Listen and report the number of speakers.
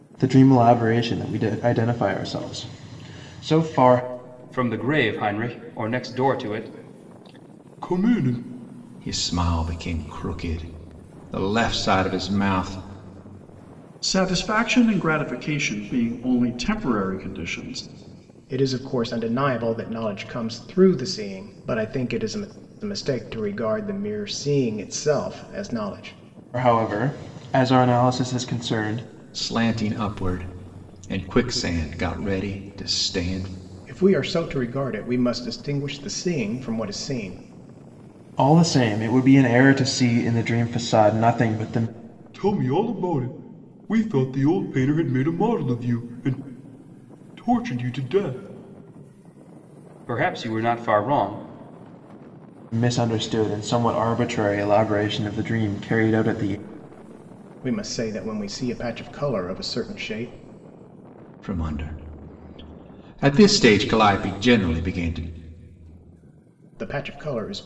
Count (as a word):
five